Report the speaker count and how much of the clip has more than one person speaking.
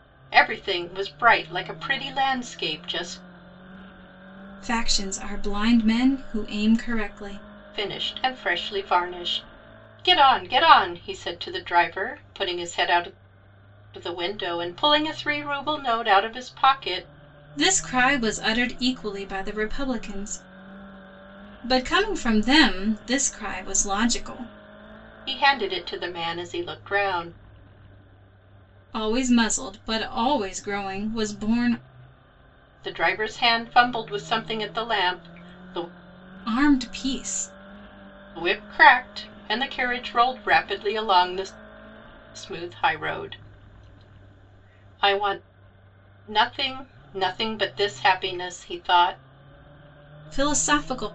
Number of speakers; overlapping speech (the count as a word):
two, no overlap